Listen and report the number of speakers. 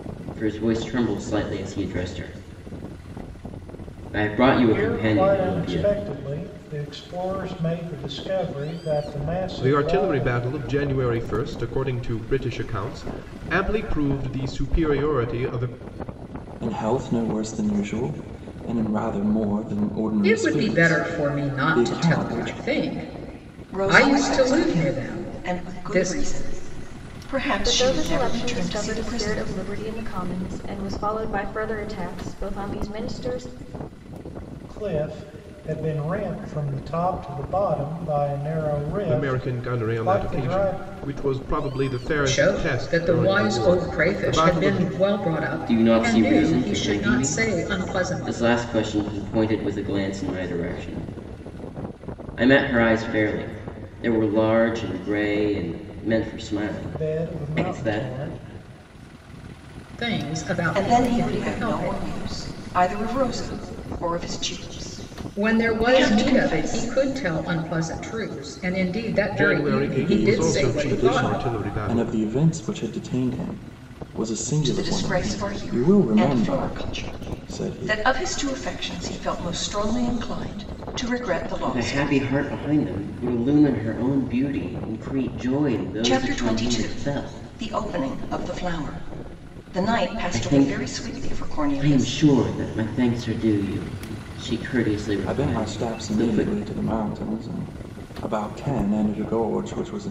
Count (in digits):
7